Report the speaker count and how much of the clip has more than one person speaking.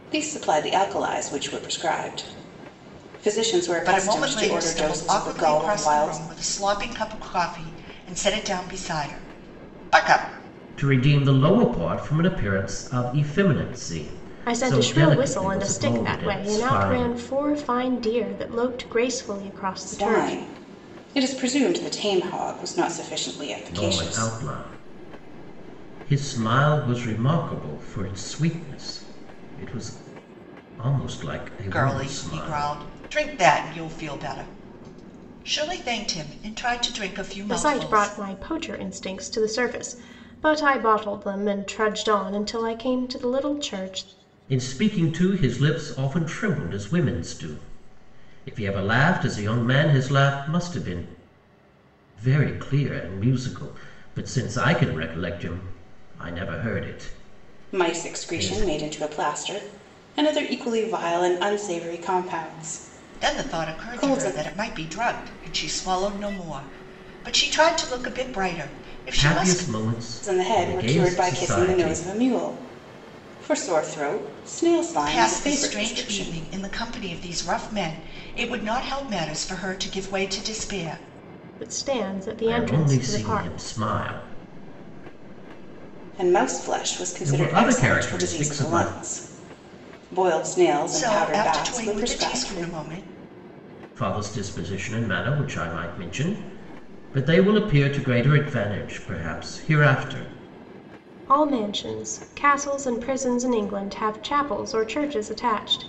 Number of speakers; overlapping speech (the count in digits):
4, about 19%